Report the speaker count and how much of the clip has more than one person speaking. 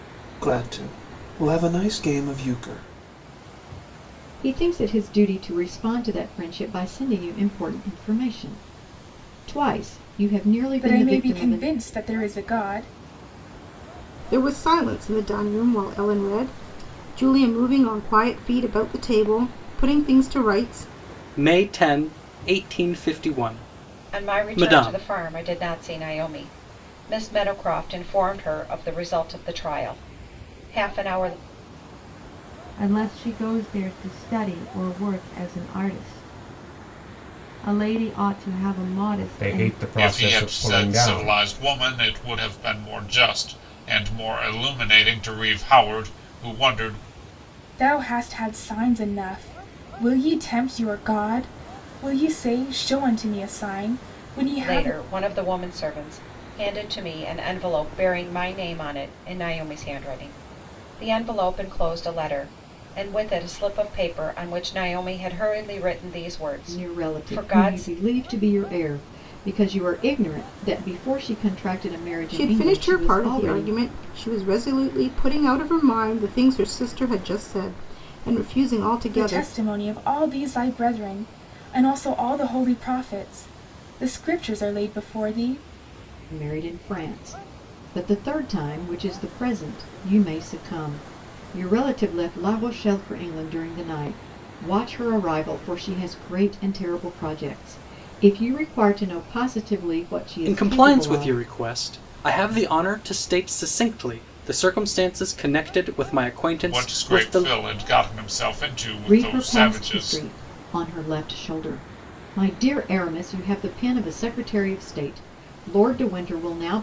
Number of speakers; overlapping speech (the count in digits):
9, about 9%